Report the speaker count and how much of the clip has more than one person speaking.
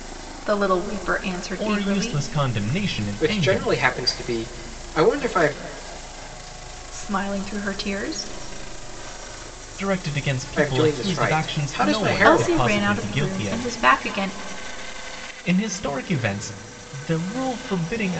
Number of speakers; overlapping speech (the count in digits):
3, about 24%